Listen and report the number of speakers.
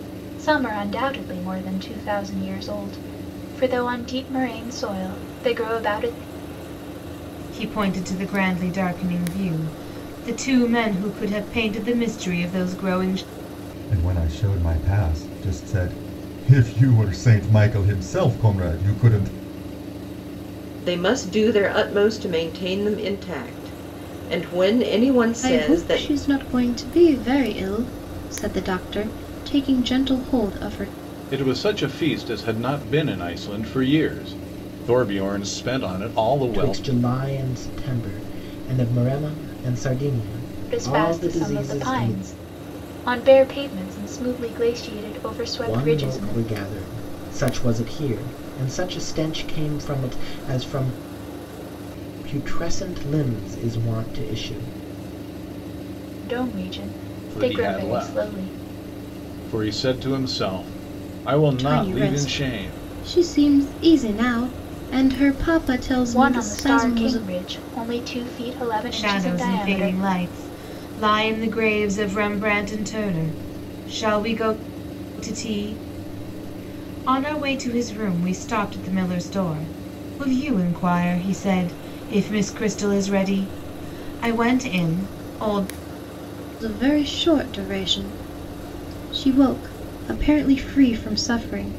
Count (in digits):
7